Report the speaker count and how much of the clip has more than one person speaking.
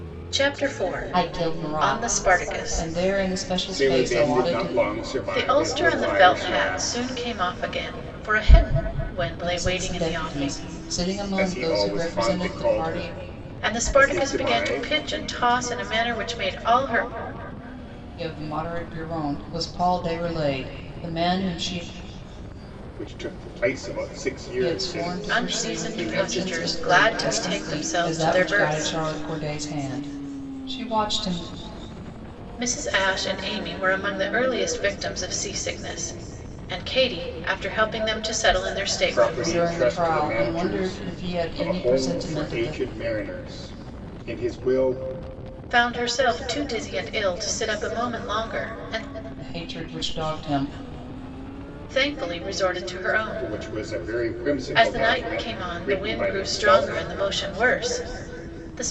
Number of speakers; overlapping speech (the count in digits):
3, about 34%